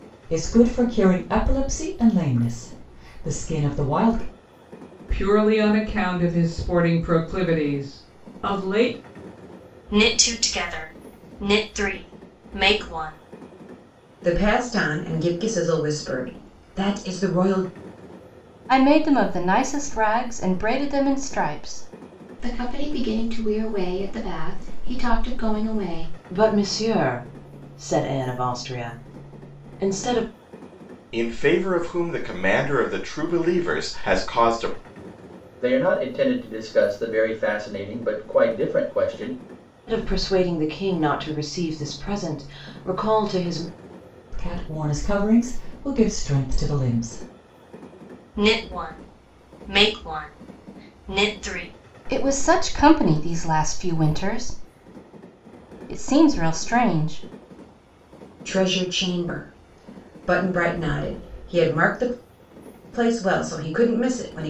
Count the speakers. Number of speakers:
nine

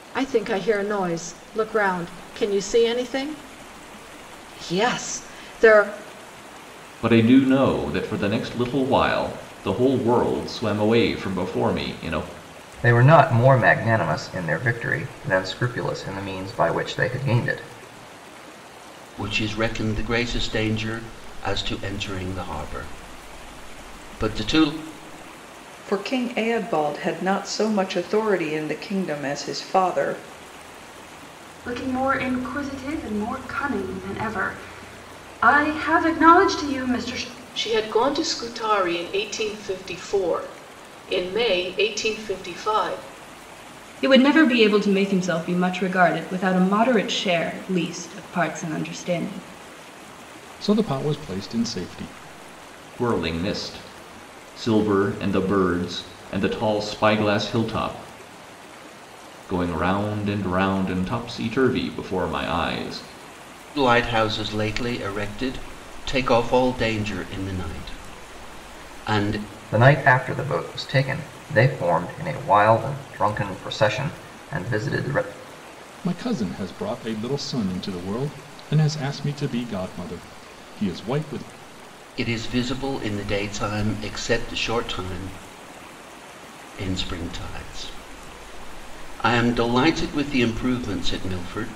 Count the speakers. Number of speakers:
nine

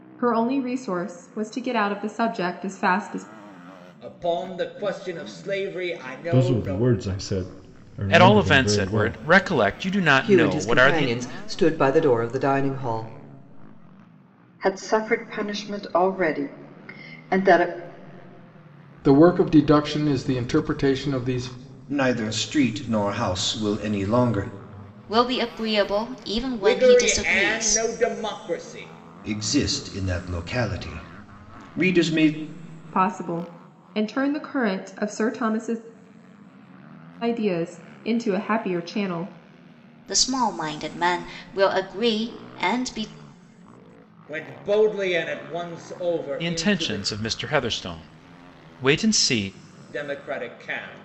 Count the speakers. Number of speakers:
nine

